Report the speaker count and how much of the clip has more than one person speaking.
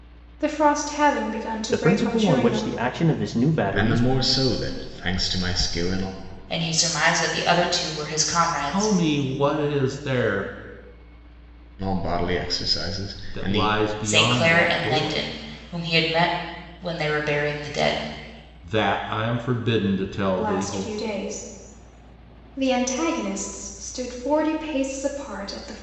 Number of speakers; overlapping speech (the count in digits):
5, about 15%